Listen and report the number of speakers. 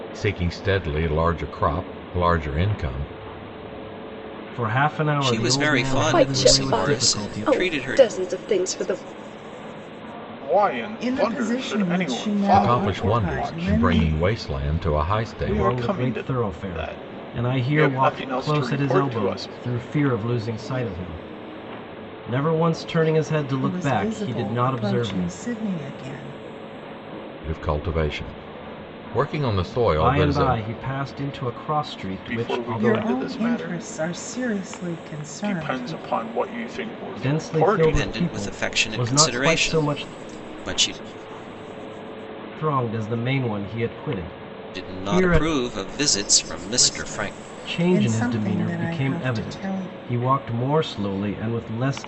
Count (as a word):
six